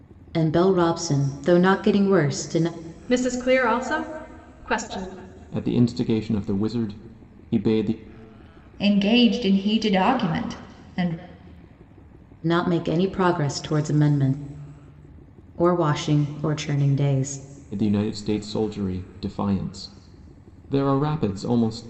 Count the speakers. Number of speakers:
four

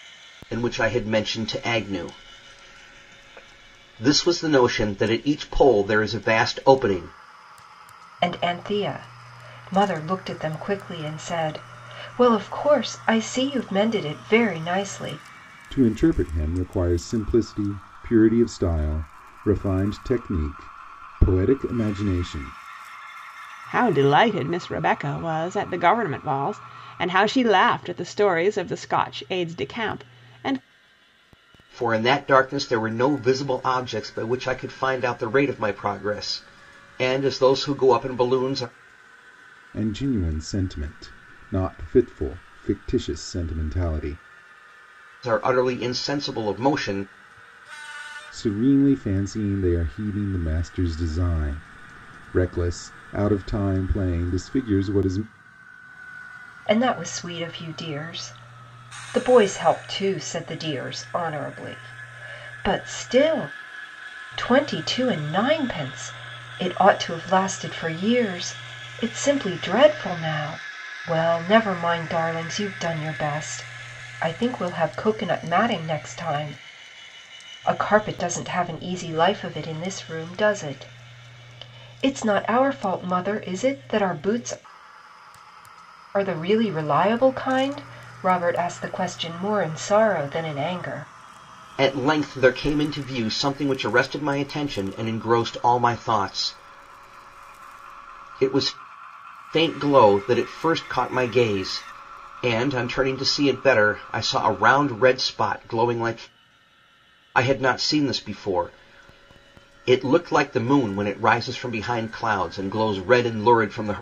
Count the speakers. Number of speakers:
four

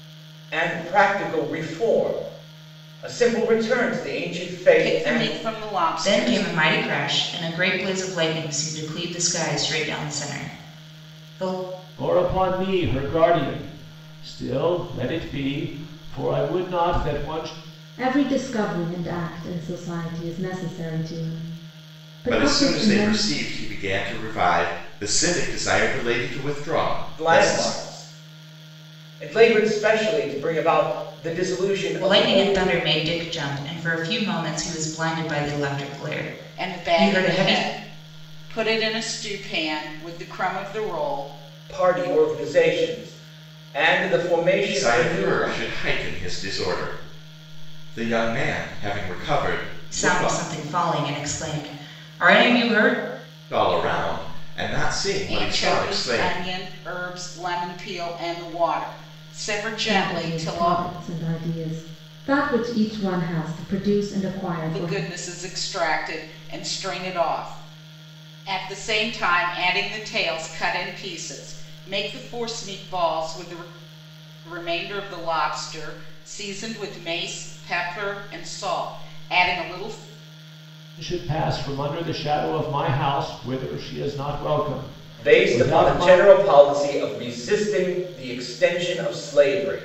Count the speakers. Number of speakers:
six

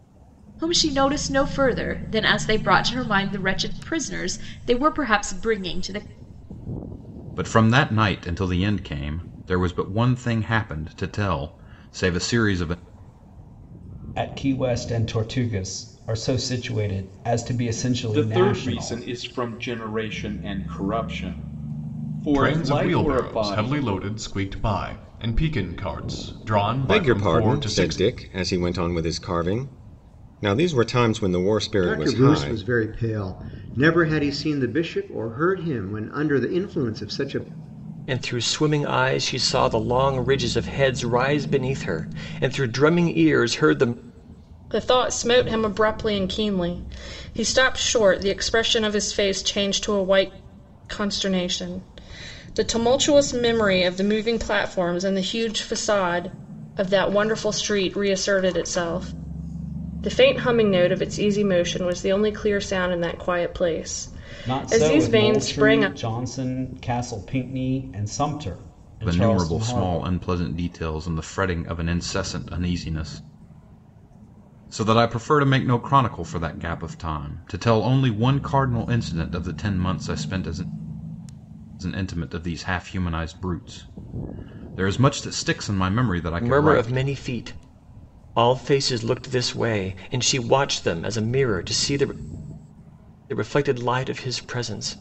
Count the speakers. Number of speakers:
nine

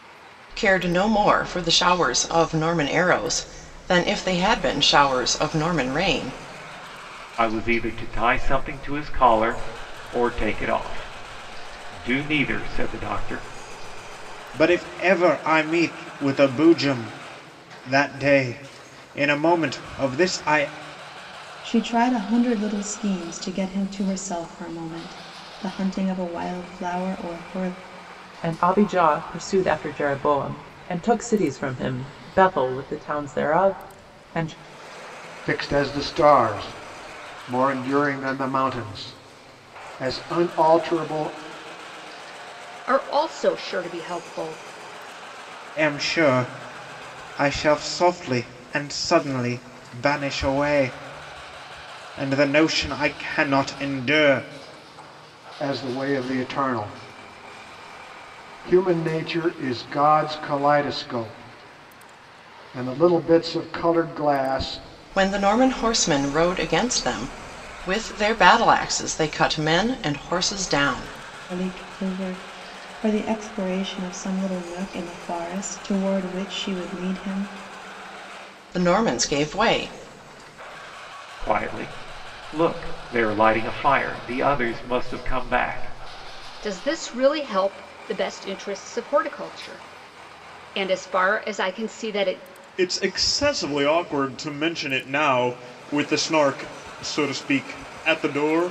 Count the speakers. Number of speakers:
seven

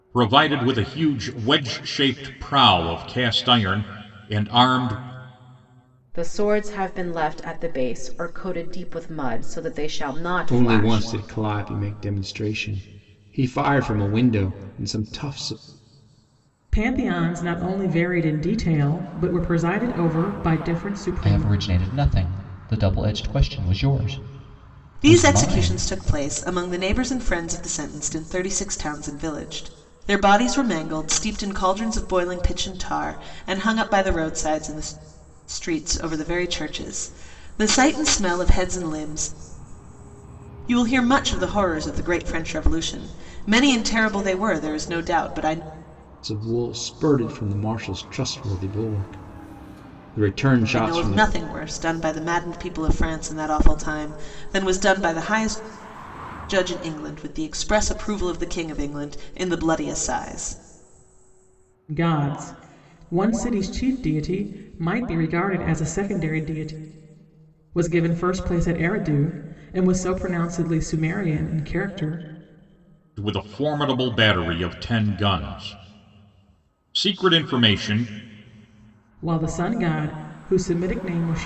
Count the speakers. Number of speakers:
six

